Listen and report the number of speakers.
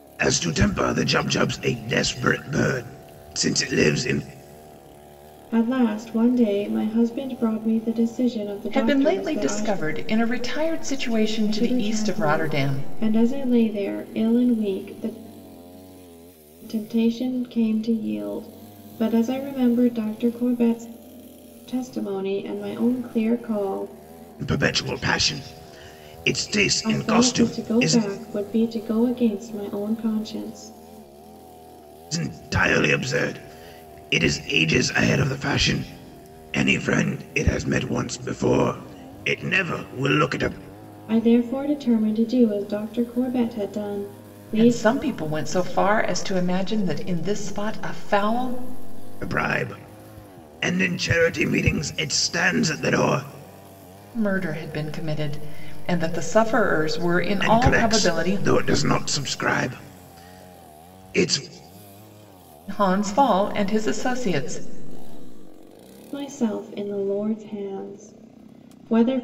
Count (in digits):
3